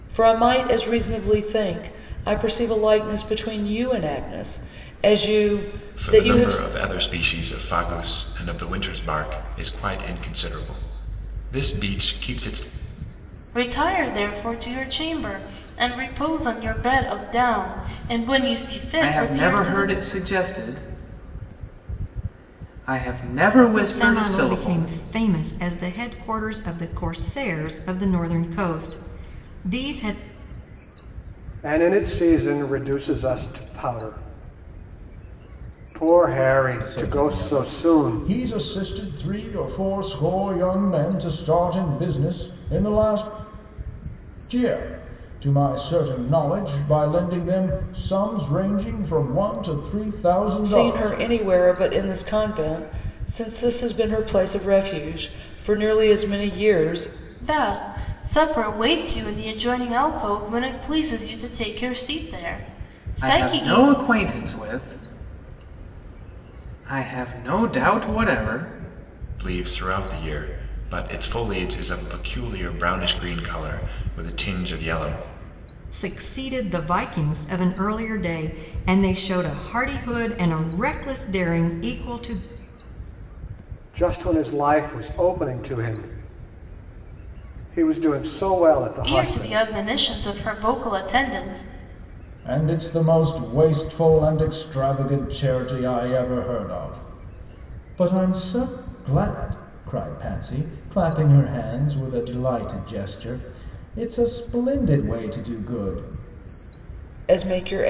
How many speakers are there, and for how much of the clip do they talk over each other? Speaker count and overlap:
7, about 6%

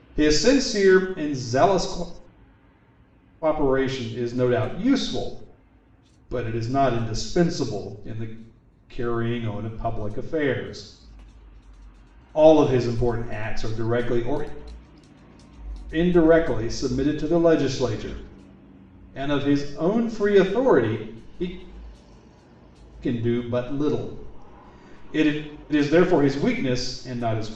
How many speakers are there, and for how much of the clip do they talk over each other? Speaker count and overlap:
1, no overlap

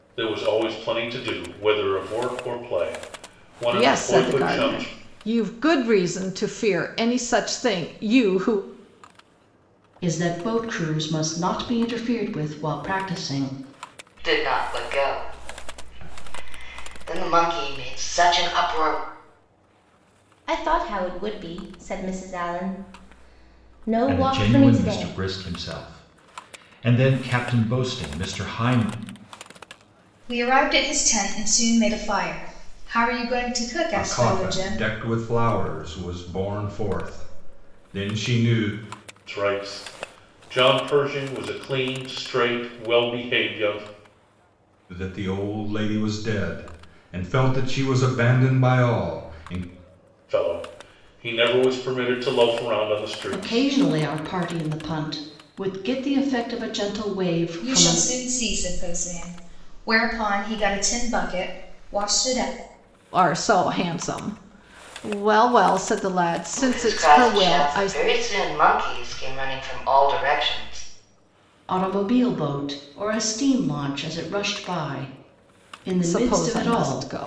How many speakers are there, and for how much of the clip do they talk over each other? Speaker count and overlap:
8, about 8%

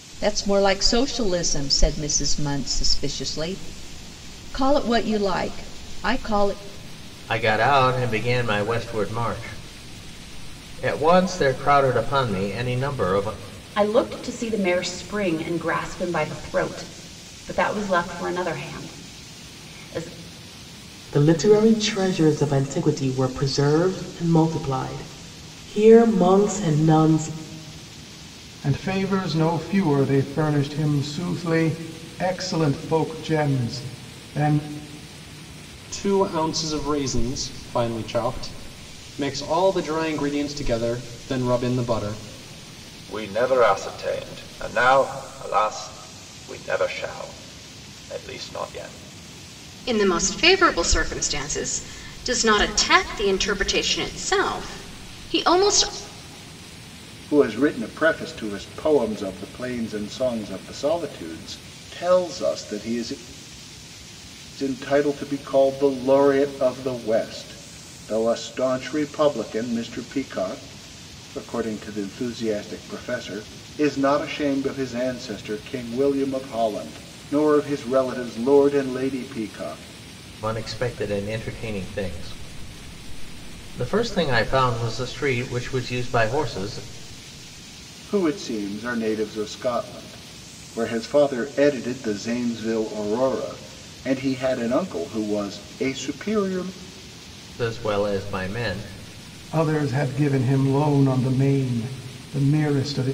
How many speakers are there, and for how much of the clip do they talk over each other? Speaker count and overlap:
9, no overlap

